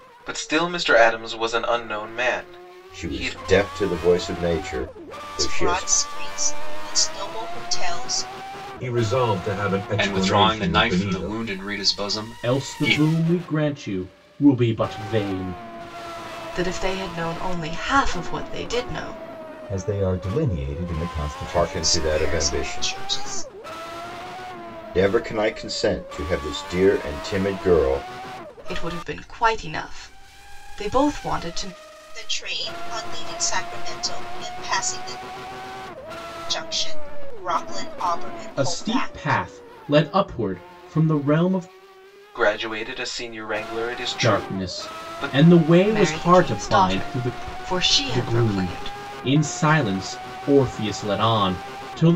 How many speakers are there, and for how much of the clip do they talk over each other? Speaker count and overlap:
8, about 17%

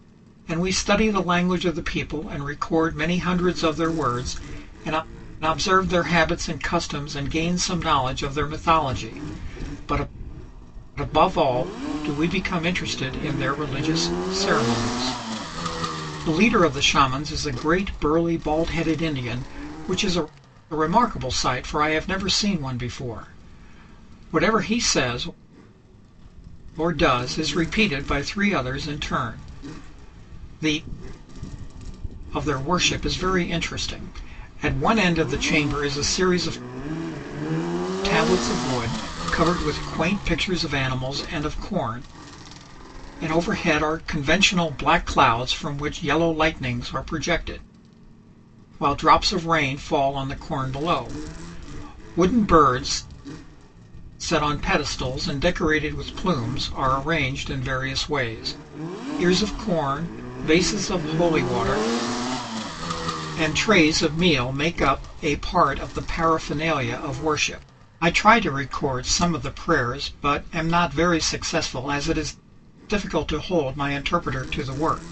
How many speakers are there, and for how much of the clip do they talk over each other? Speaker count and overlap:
1, no overlap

